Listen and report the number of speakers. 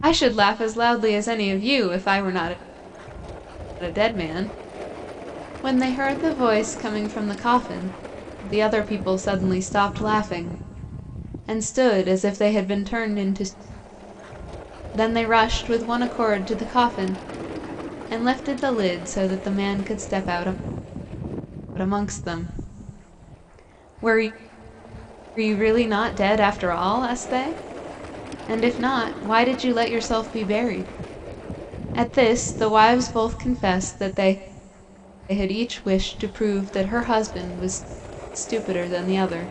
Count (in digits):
1